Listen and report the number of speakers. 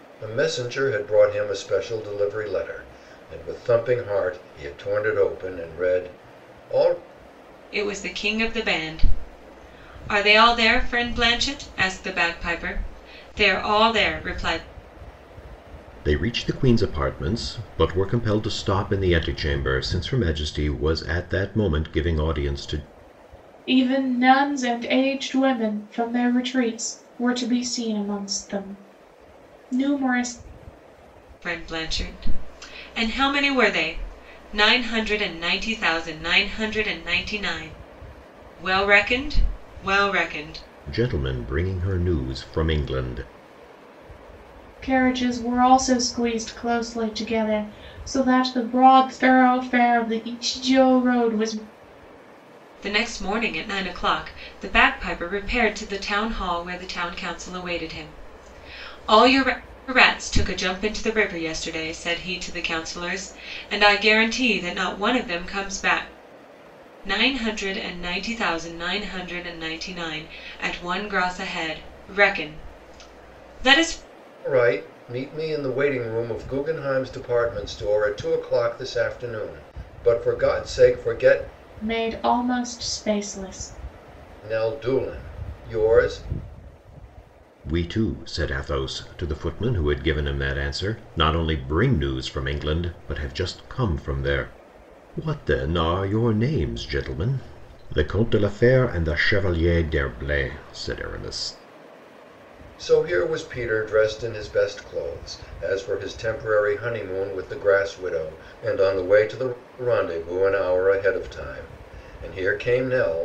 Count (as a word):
four